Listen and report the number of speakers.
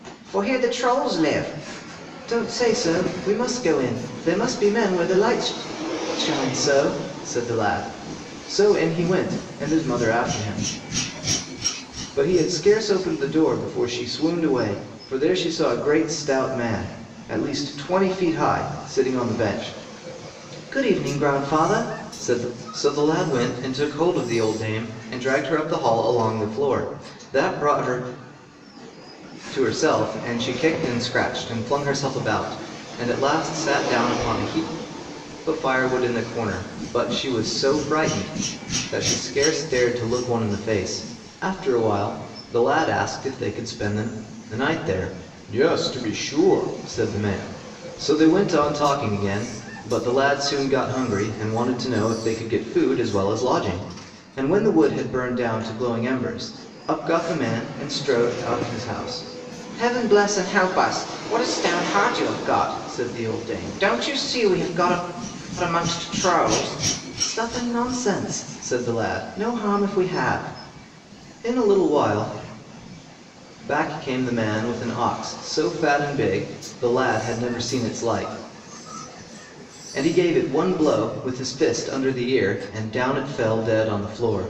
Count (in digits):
1